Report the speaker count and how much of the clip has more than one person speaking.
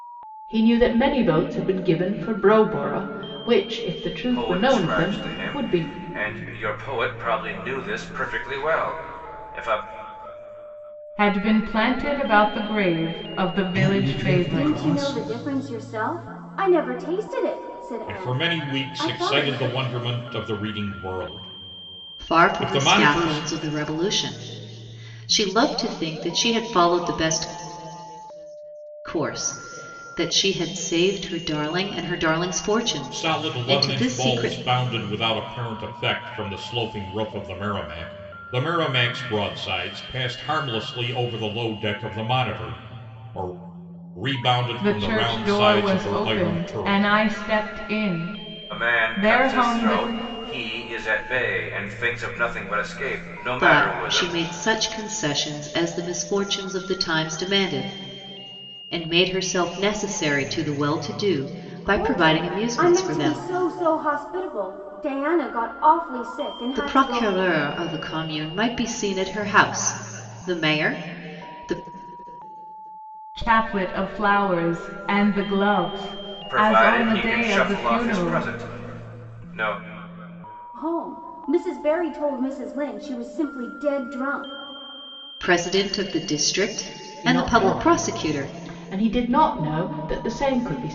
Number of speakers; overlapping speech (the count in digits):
7, about 20%